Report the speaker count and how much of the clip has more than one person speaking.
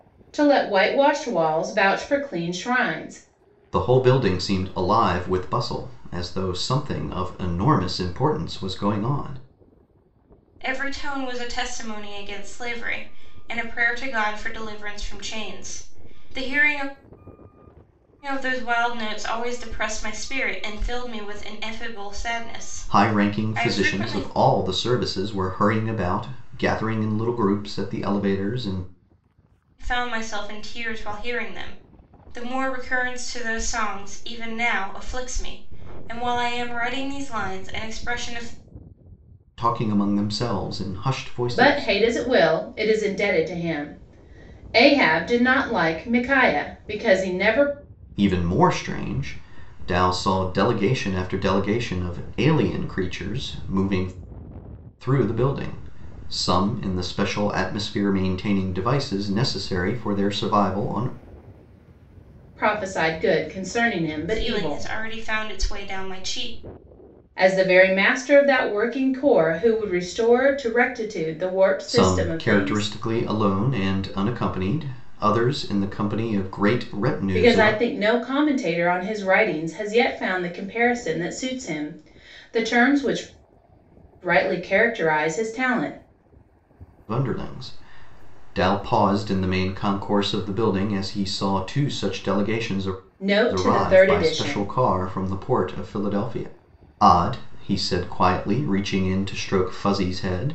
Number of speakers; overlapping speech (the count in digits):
3, about 5%